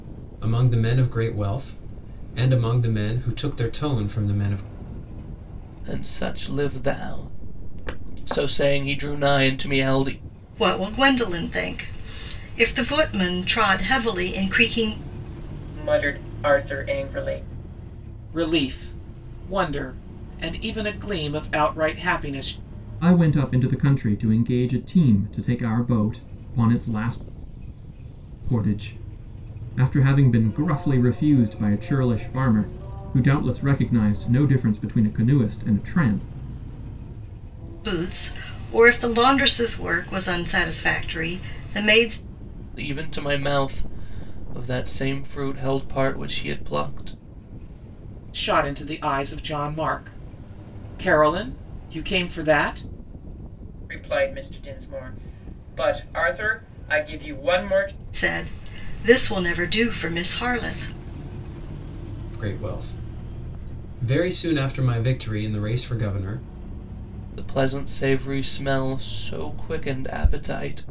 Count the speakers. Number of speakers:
6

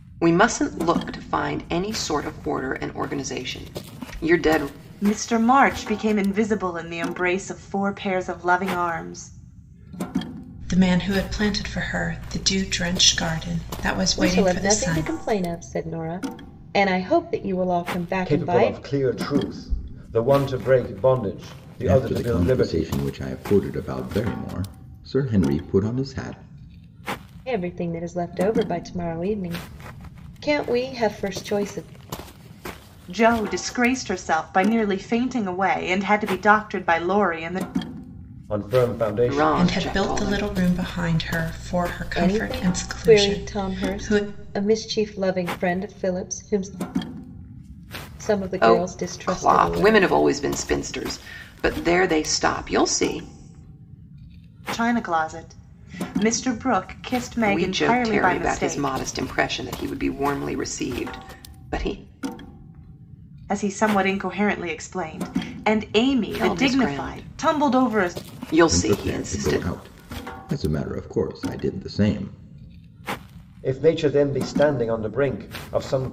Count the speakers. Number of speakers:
6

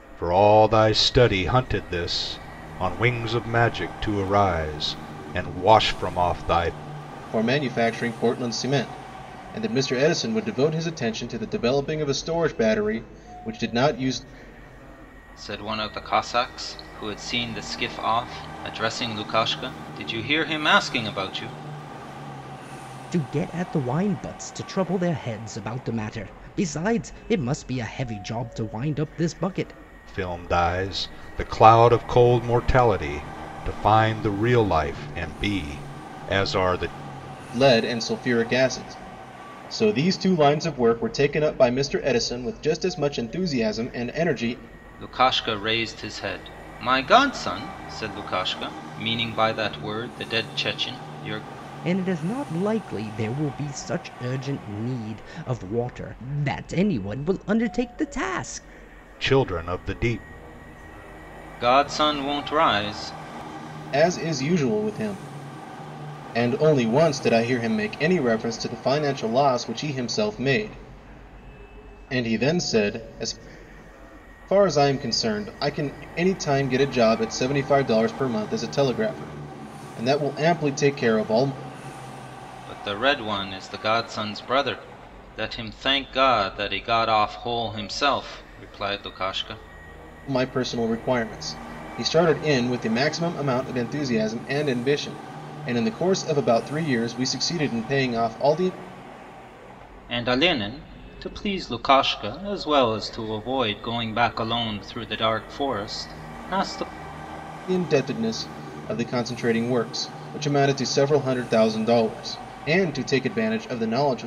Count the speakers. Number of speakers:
4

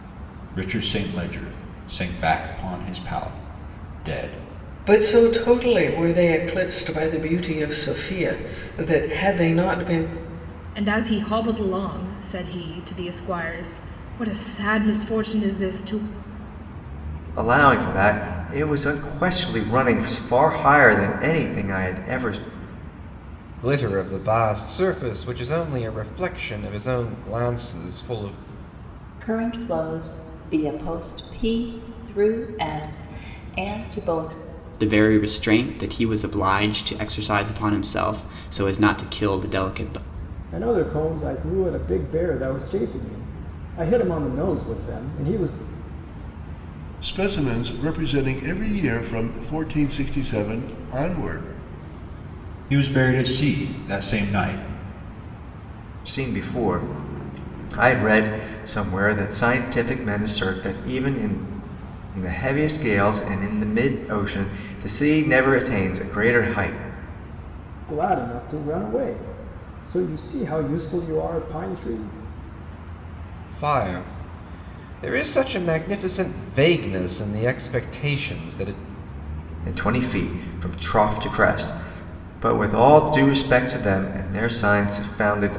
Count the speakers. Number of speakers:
9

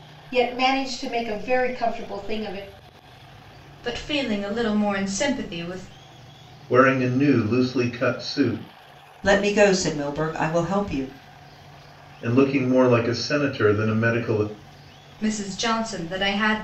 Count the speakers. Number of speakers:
4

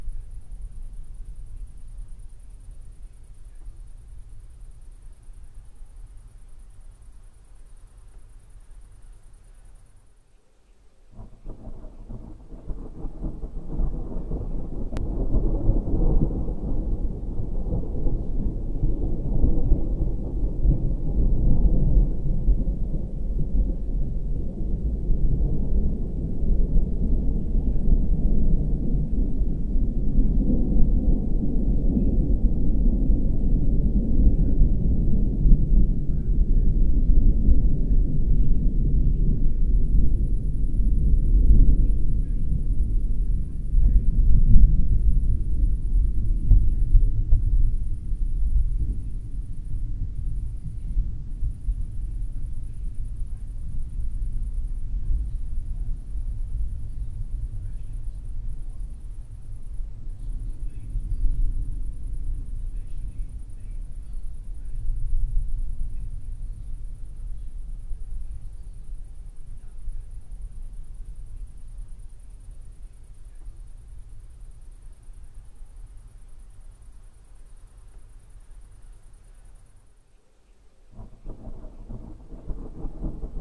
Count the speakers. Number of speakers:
0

